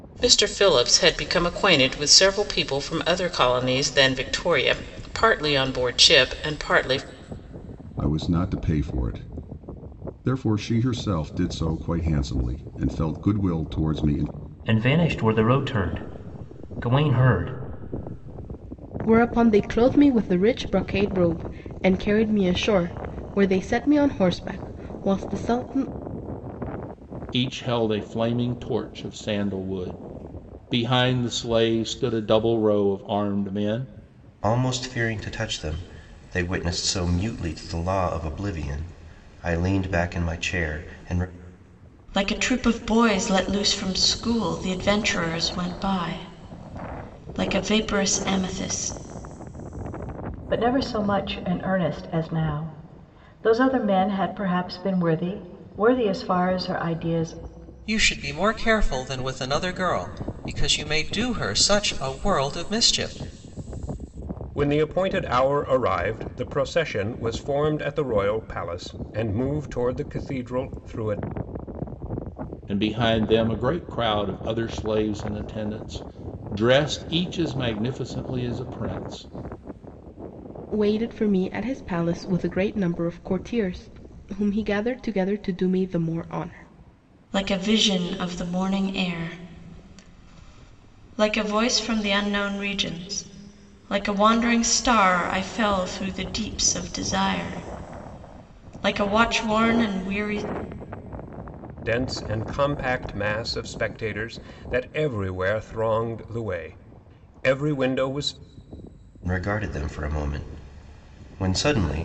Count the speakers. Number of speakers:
ten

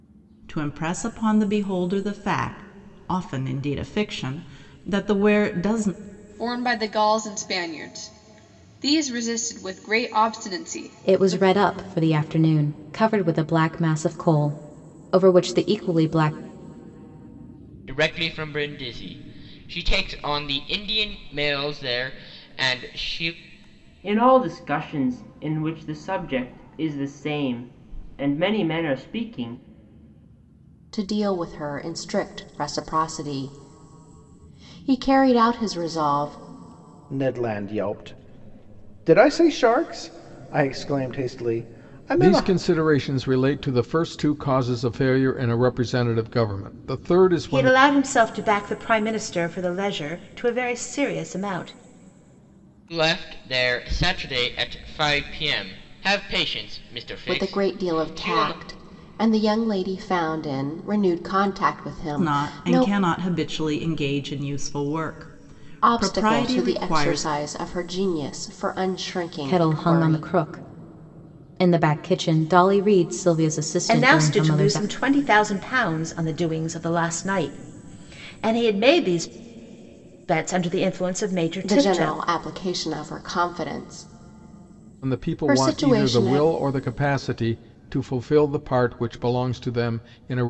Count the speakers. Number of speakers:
nine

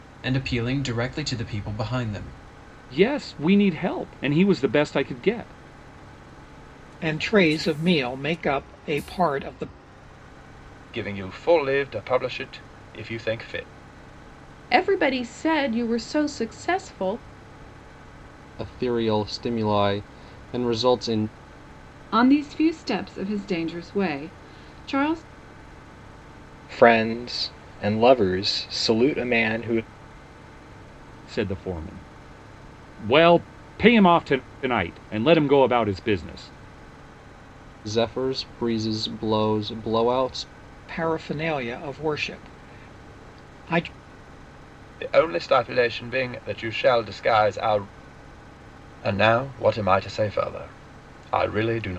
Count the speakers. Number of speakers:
eight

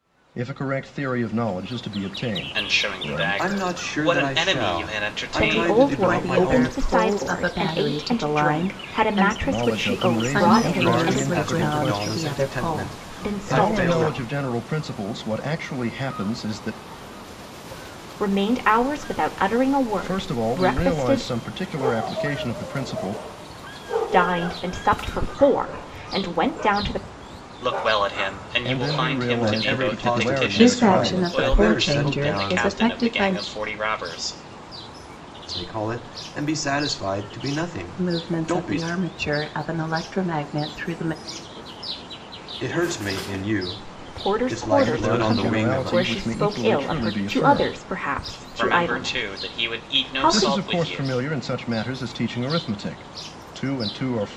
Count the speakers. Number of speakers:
five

